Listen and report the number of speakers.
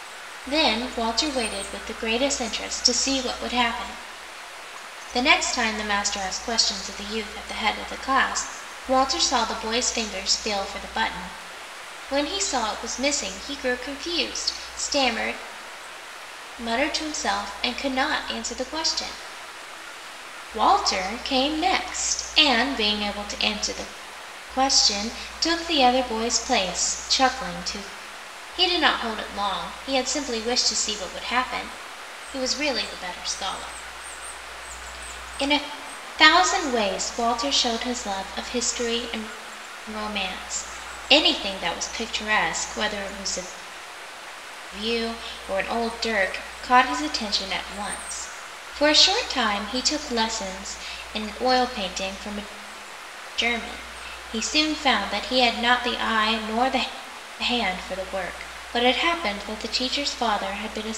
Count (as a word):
one